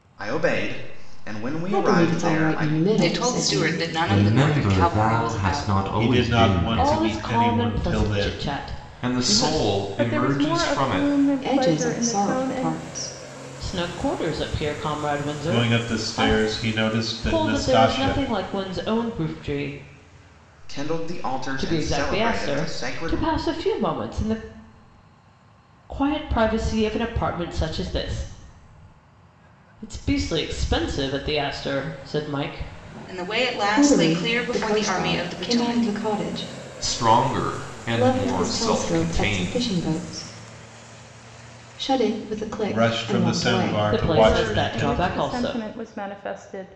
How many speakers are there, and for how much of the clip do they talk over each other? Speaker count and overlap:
eight, about 44%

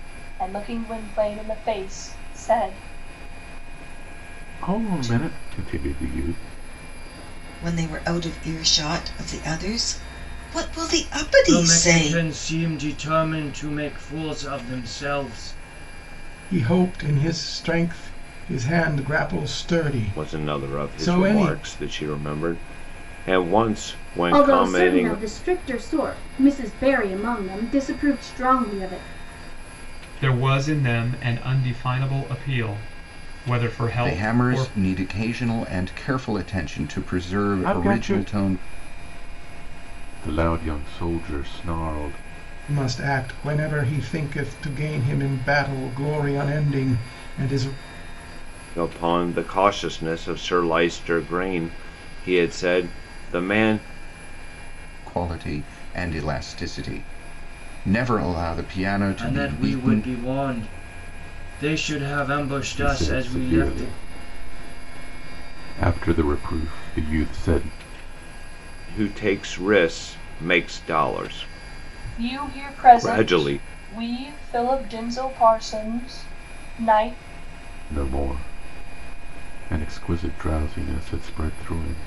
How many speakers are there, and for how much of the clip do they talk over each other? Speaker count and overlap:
nine, about 11%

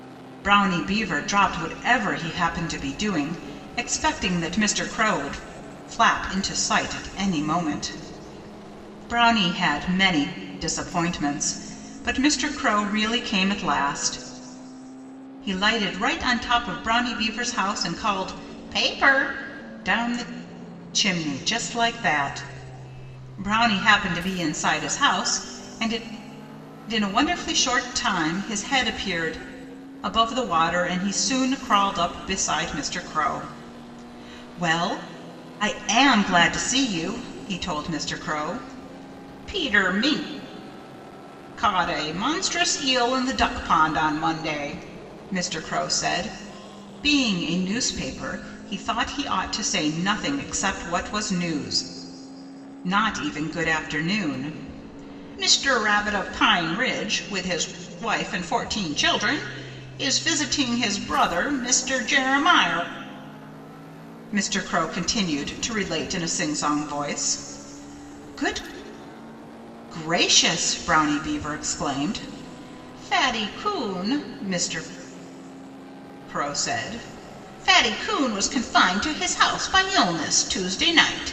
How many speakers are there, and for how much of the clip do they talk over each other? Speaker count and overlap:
one, no overlap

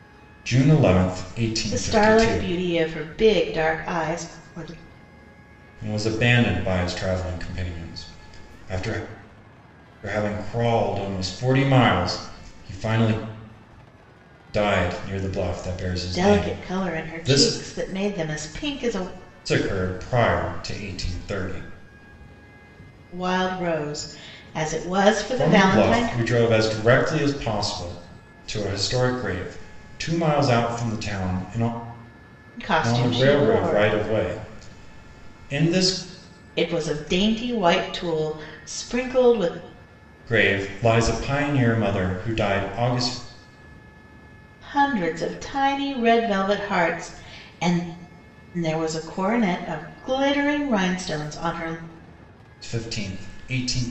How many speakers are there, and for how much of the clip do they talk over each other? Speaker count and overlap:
two, about 8%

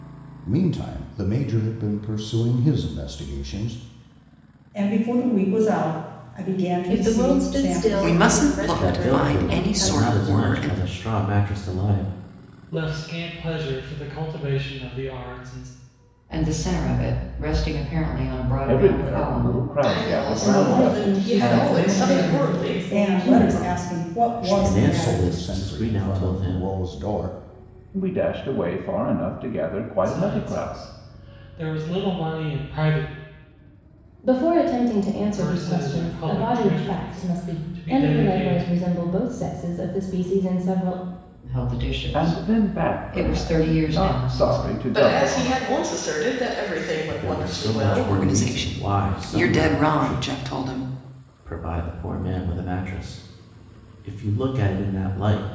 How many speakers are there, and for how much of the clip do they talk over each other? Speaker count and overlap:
ten, about 41%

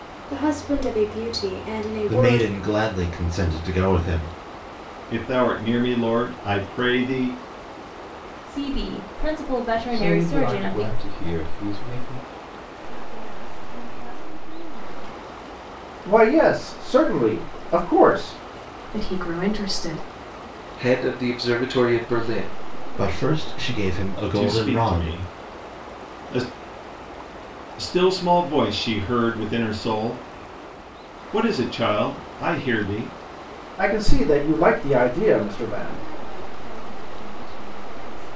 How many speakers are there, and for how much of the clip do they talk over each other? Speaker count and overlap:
nine, about 12%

